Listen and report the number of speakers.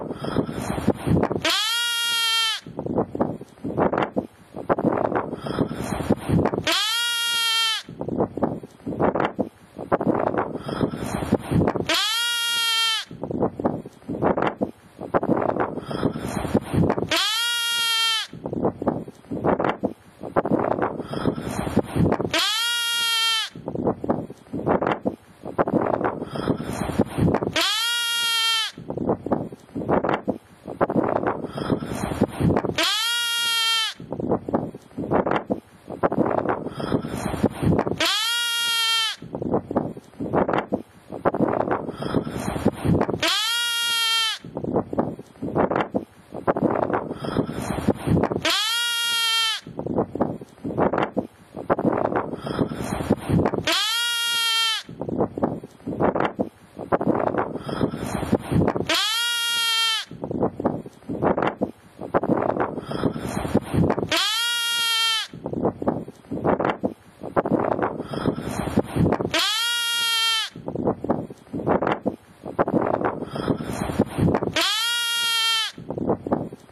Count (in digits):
0